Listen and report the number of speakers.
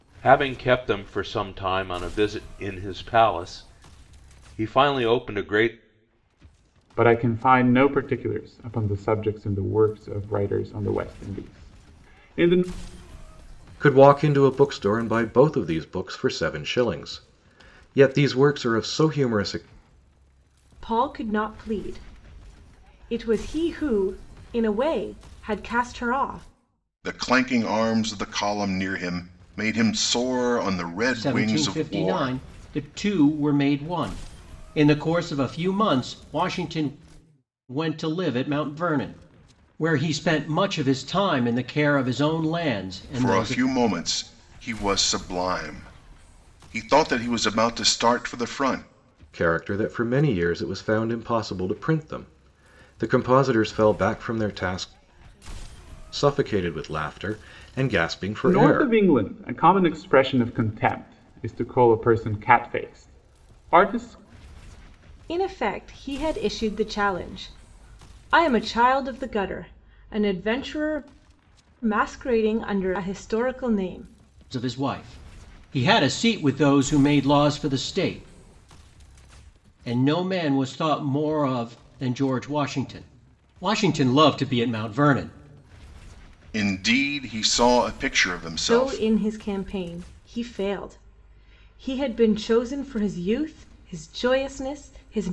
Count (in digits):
6